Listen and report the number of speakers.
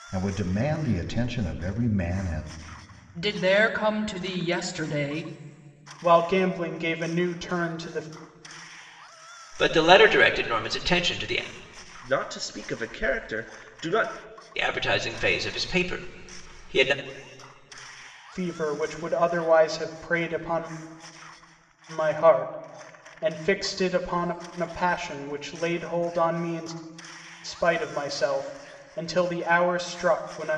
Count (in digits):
5